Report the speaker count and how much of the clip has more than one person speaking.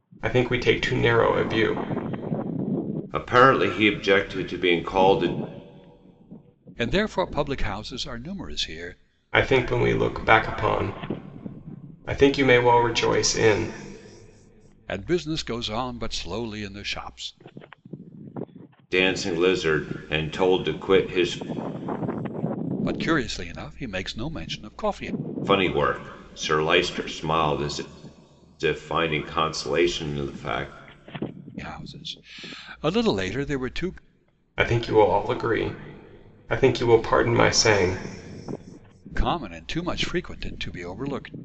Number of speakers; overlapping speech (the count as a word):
three, no overlap